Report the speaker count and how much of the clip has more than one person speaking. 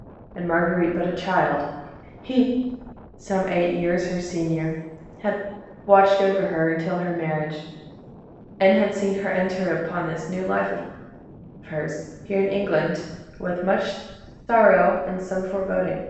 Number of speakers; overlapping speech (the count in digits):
1, no overlap